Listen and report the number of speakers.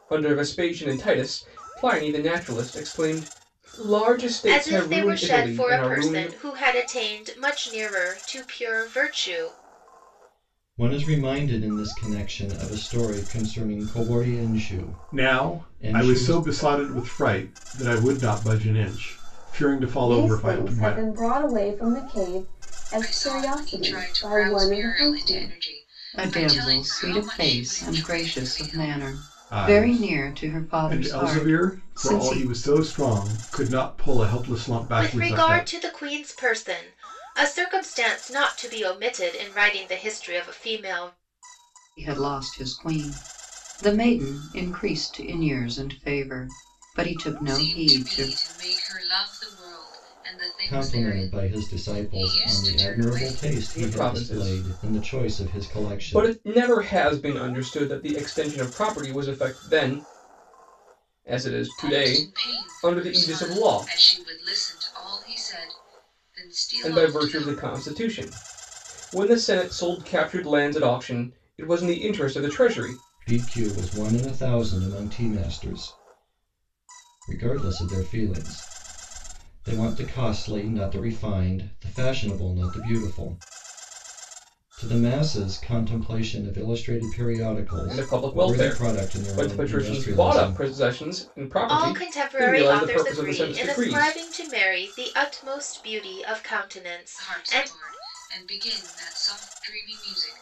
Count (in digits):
7